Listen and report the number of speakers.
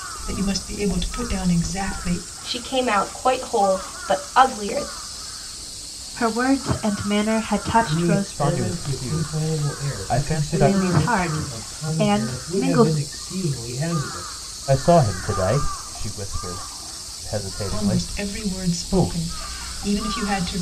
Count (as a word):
five